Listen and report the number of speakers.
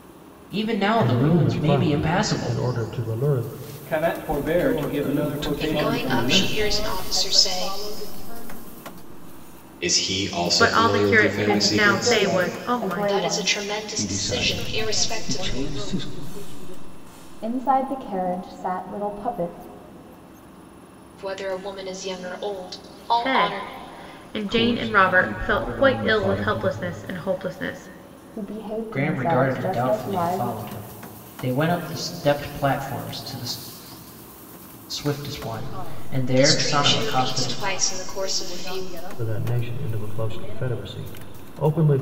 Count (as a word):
nine